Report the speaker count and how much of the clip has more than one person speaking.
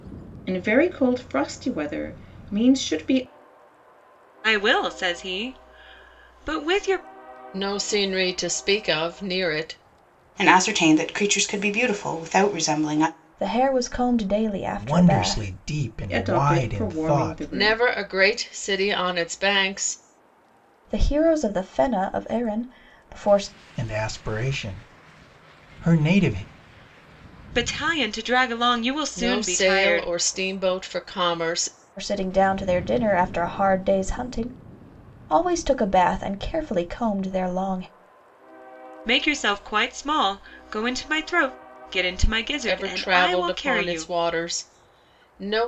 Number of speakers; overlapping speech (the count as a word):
six, about 11%